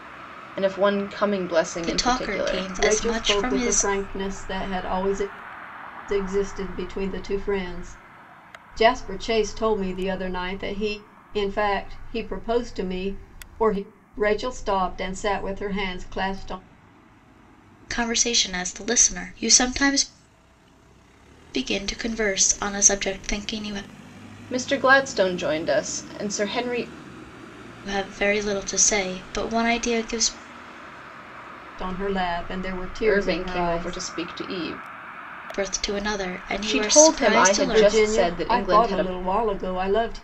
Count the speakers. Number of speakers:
3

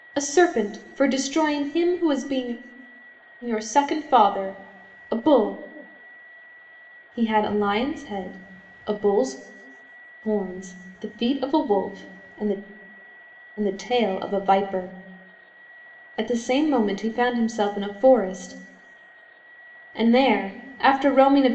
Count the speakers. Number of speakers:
1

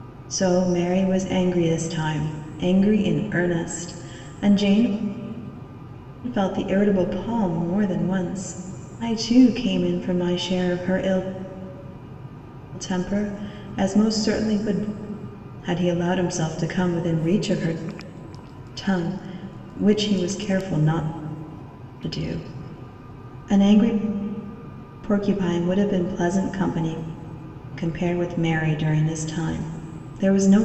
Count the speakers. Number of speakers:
1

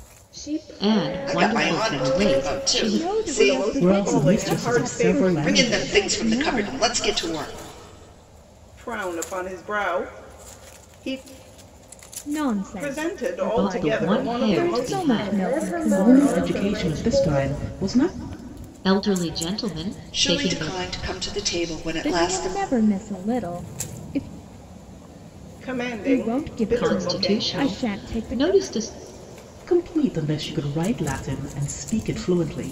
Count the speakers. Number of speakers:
6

